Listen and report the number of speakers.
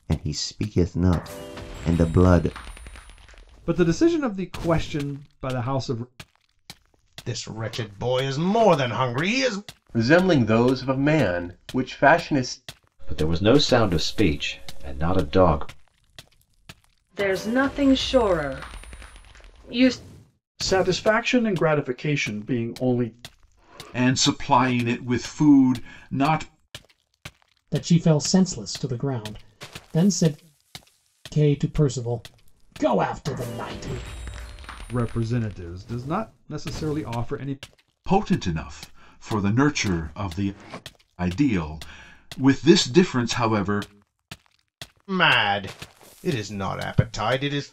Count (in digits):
9